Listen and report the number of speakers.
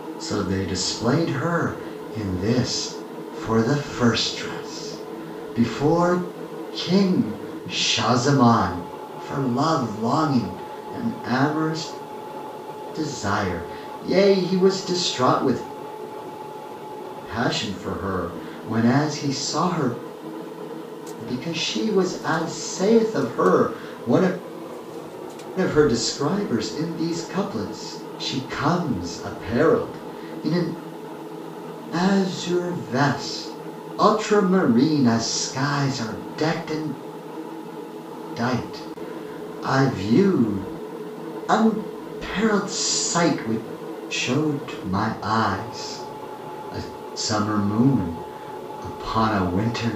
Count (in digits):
1